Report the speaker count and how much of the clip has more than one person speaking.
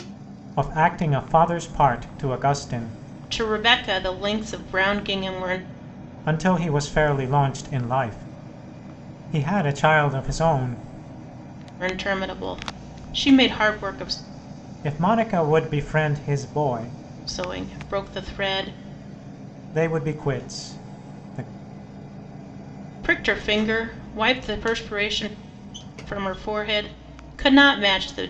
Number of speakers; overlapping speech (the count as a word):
two, no overlap